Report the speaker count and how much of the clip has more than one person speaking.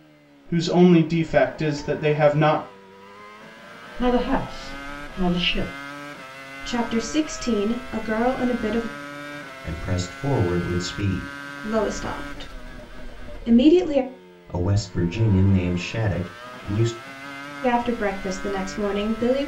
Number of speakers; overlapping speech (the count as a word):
four, no overlap